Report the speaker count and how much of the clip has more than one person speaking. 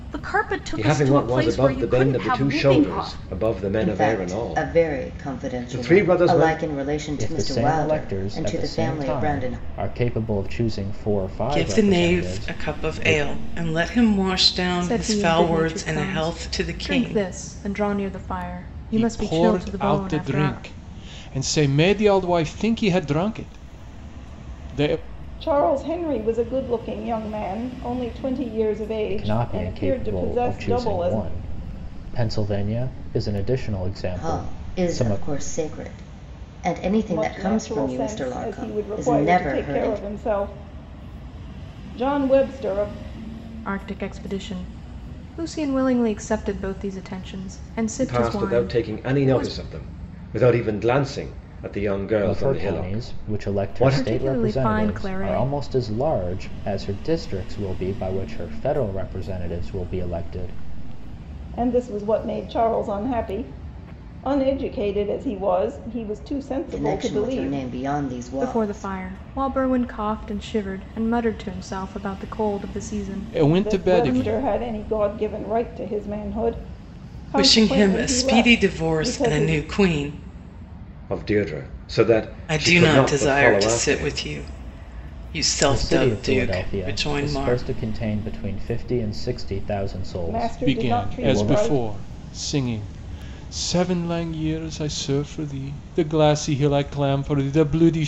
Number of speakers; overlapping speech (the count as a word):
eight, about 36%